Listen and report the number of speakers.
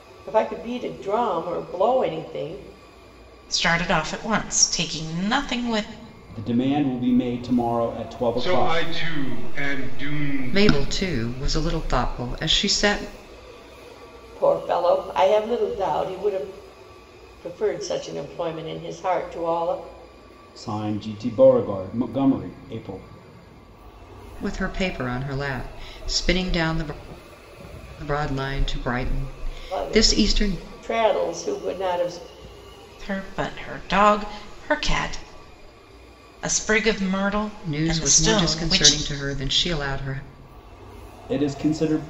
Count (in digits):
5